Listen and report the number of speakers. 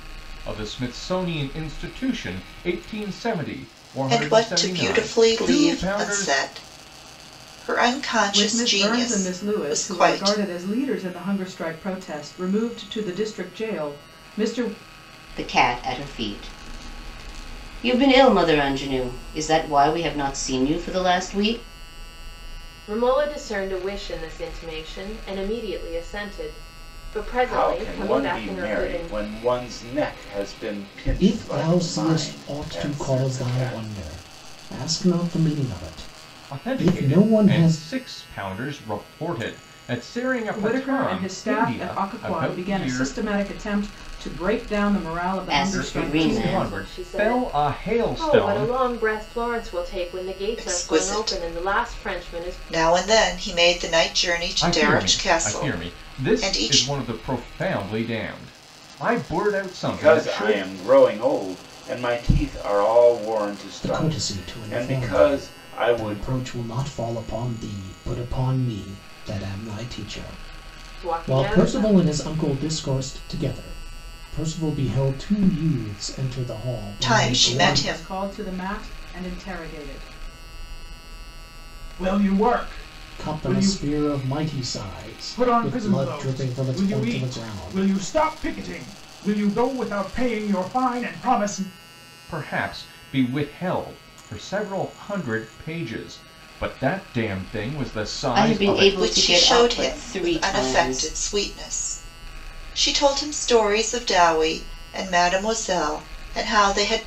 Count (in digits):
7